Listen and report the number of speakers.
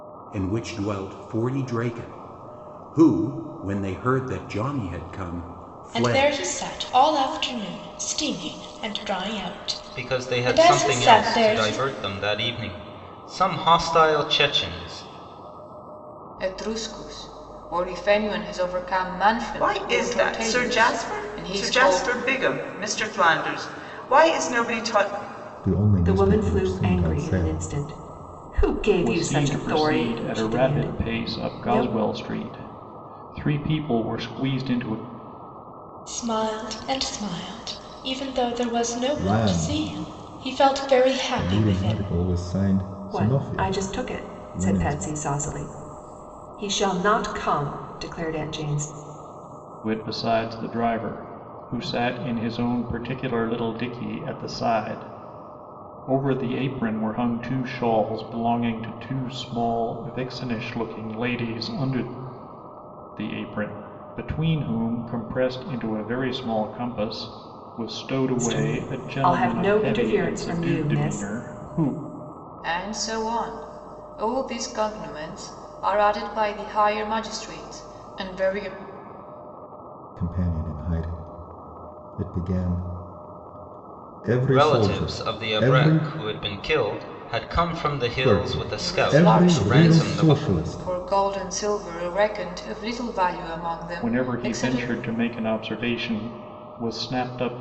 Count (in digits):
8